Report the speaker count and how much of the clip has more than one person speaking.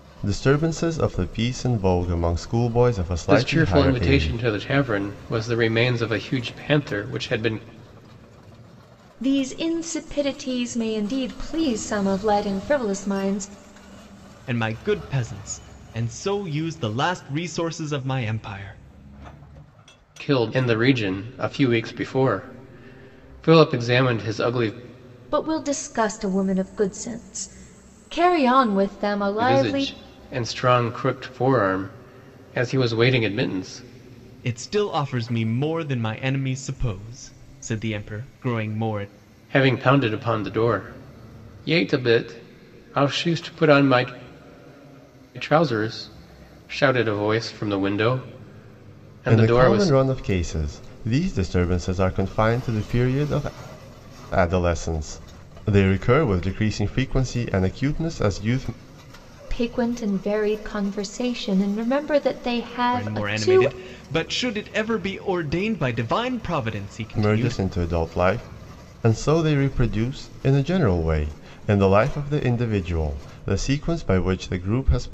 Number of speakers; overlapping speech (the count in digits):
4, about 5%